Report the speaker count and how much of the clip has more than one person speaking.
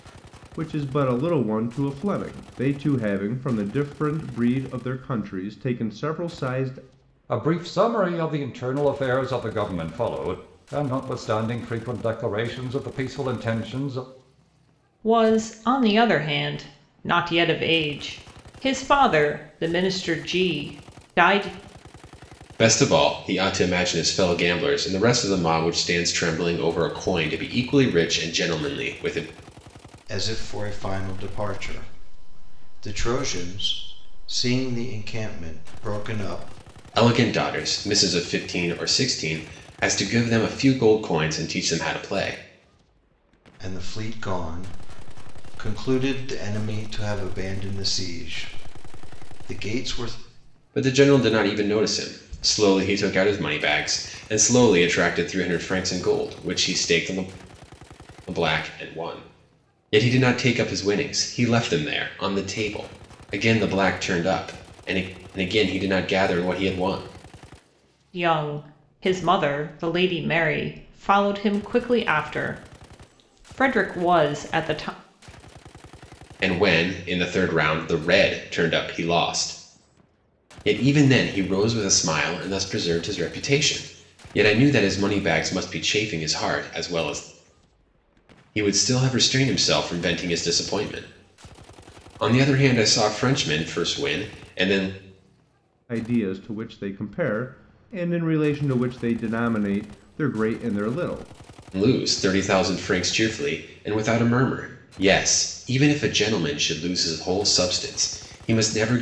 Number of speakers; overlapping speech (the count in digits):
5, no overlap